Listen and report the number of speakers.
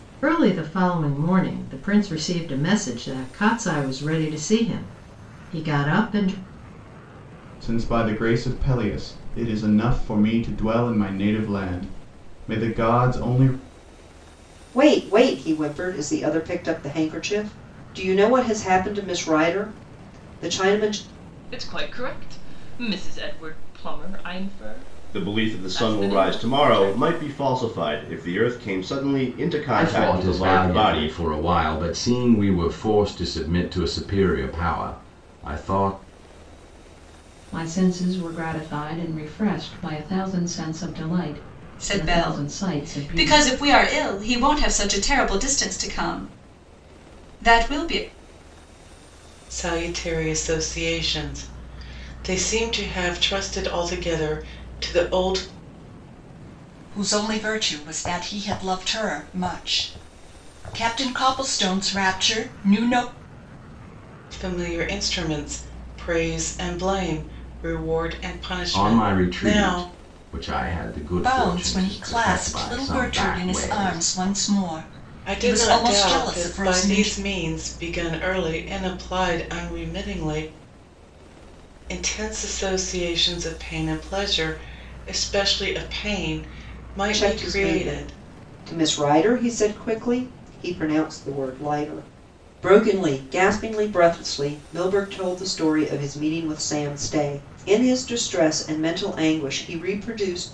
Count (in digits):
10